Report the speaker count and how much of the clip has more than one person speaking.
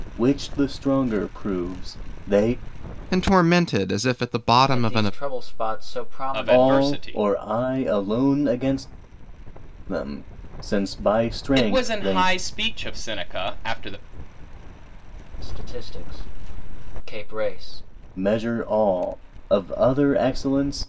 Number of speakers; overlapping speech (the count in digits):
4, about 10%